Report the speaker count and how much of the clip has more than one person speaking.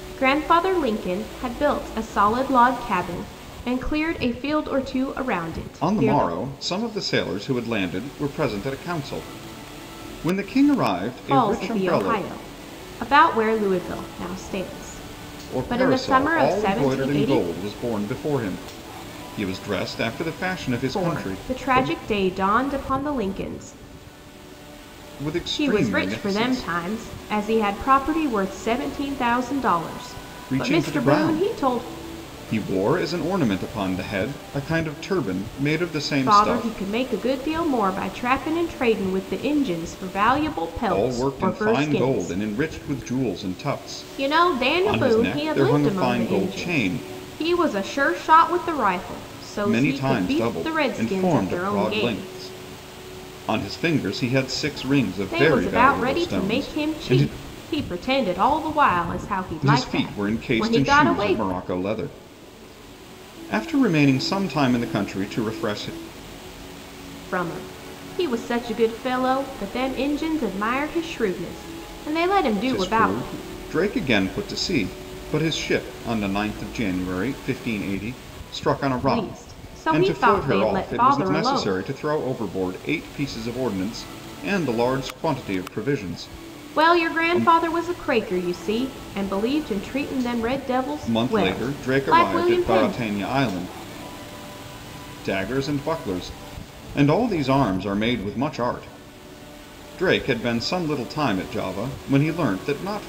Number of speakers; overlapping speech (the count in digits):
2, about 24%